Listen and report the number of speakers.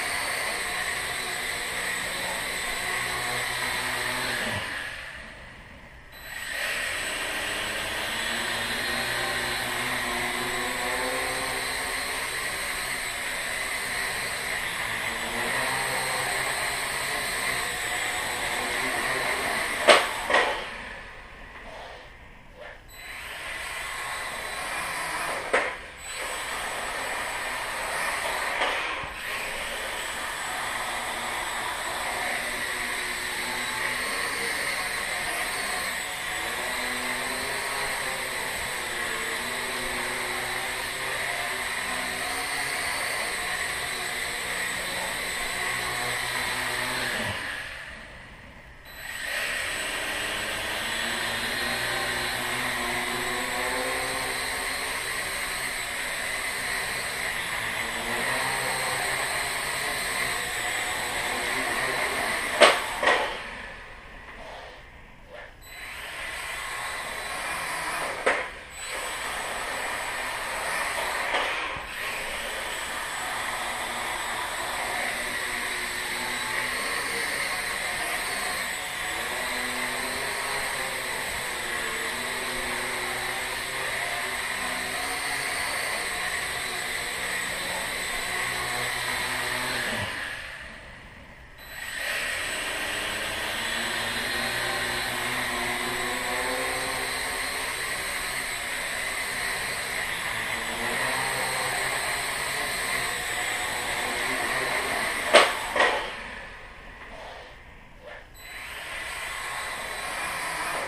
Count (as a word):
zero